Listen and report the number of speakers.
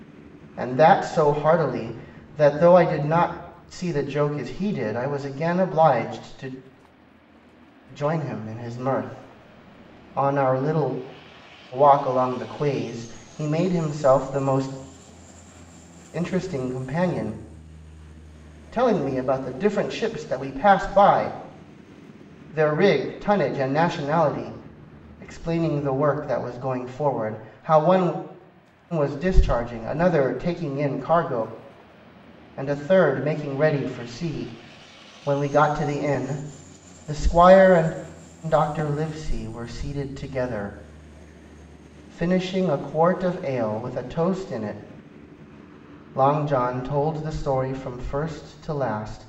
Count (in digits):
1